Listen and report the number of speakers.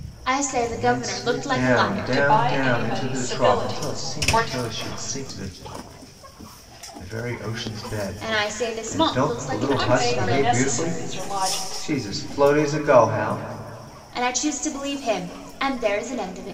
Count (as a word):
three